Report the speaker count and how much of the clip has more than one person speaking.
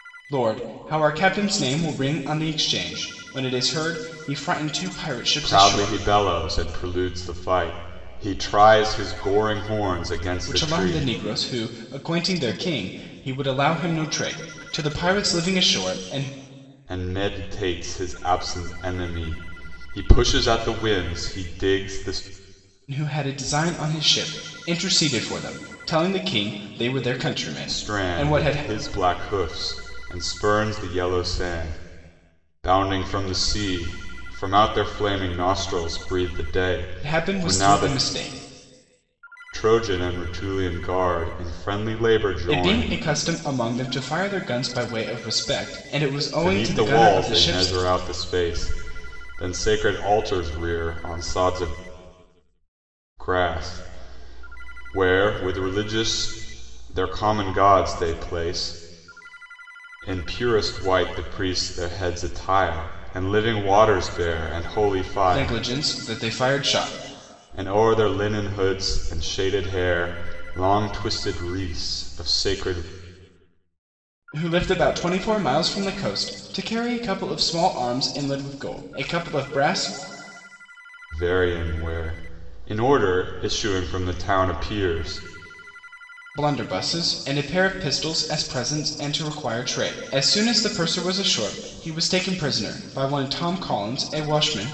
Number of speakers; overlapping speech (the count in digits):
2, about 6%